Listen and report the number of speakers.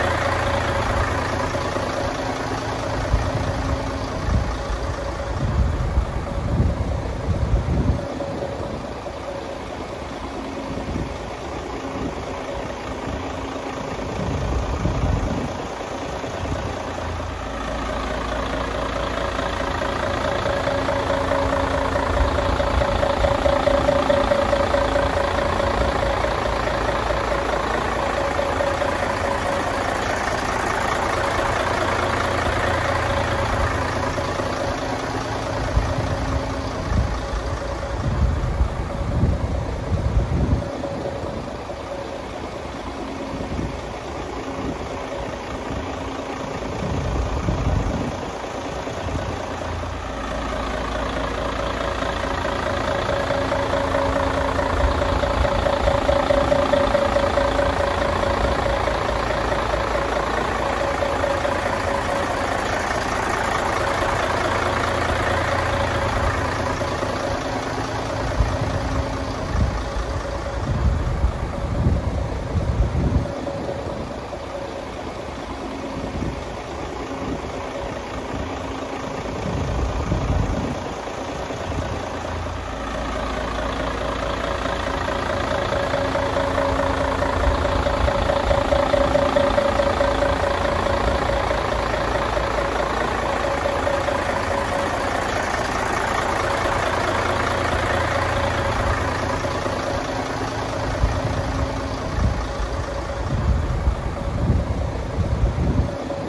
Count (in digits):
0